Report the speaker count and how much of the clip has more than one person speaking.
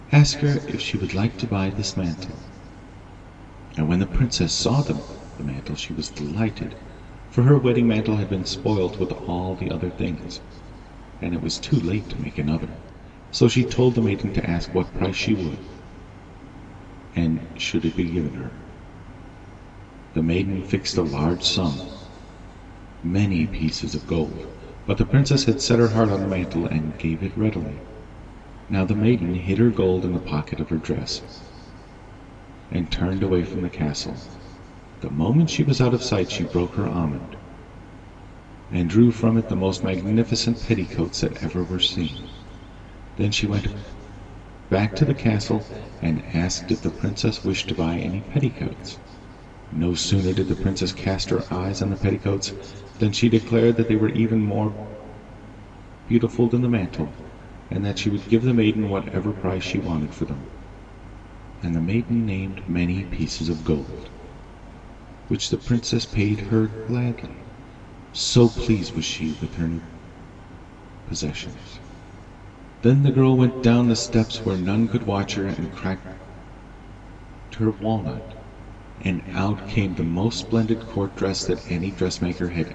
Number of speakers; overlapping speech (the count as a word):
one, no overlap